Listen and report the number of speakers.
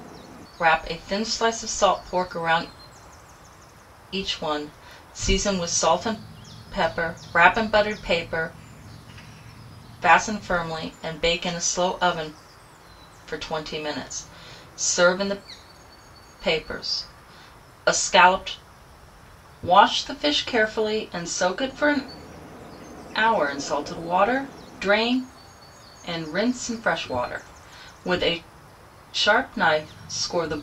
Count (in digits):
1